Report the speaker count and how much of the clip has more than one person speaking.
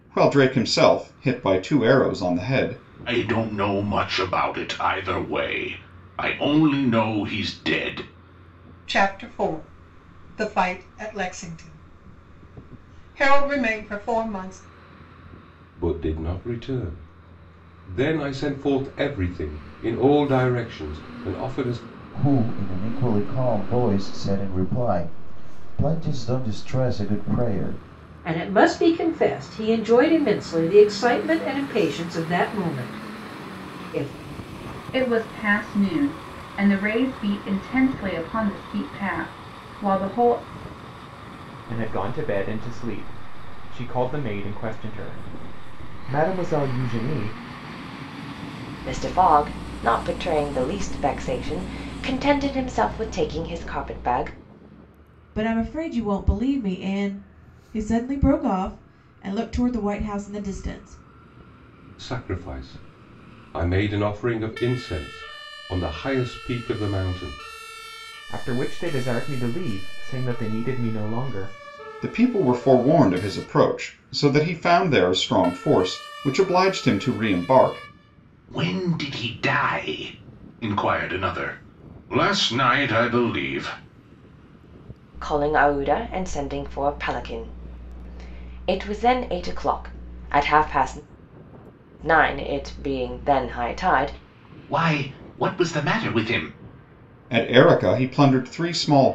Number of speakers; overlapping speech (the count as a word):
ten, no overlap